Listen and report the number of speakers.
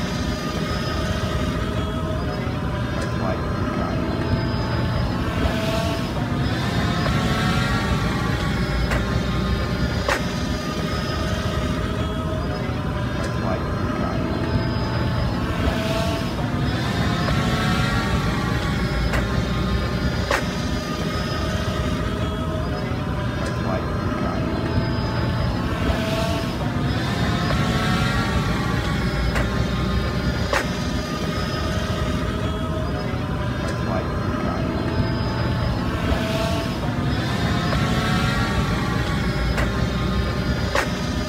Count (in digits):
0